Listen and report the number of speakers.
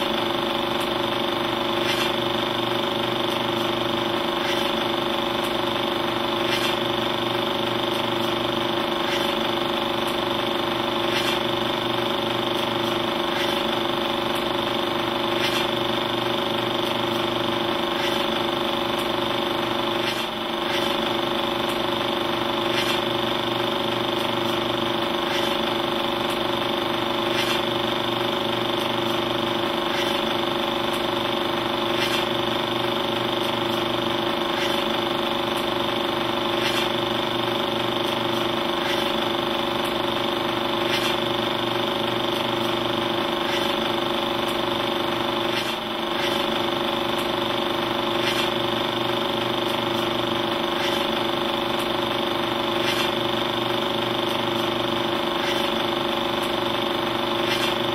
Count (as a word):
zero